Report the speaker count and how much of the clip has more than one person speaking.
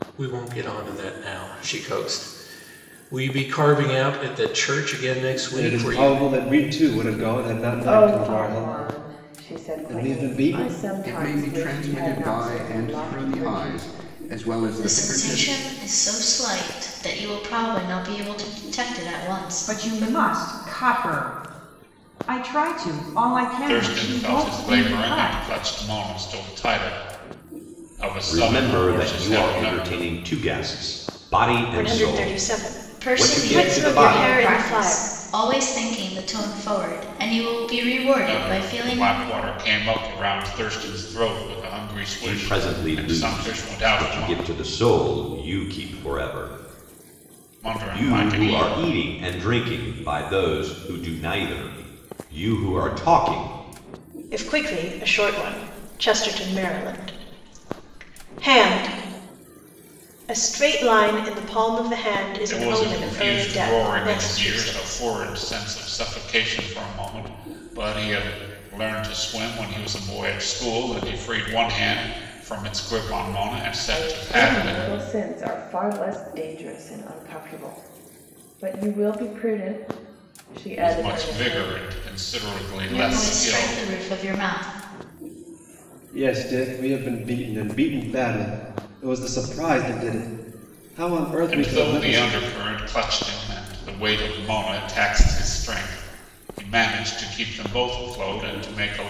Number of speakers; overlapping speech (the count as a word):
nine, about 25%